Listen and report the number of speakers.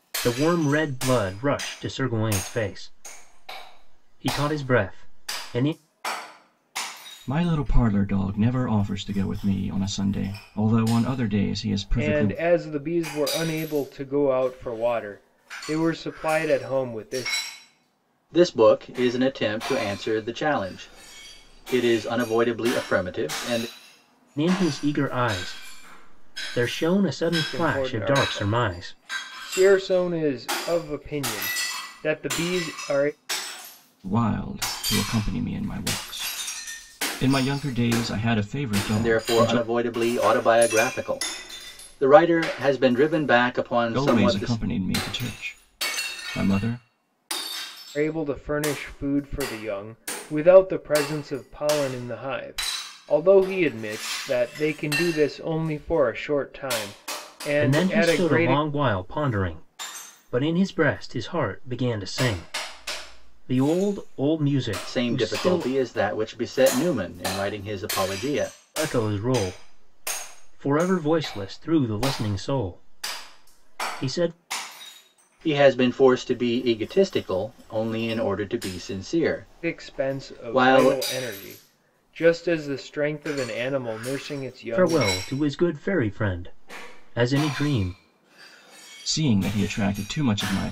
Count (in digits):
4